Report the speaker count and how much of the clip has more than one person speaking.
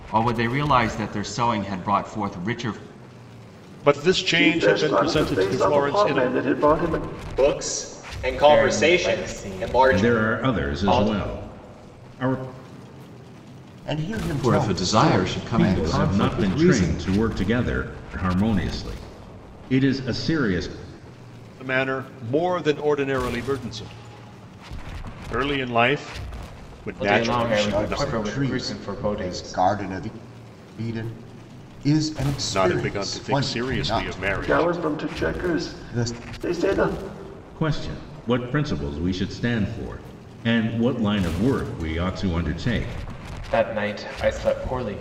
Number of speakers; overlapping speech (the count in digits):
8, about 30%